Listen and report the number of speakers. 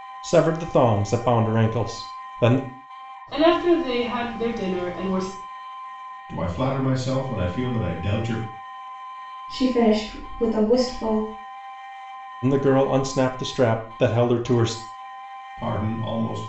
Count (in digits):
4